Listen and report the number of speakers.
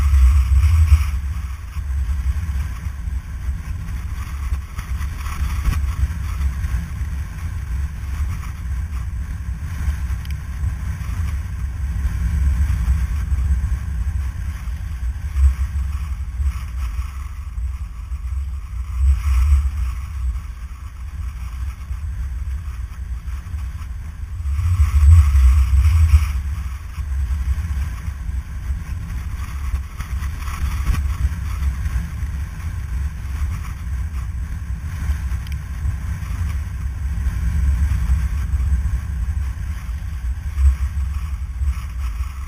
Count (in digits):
0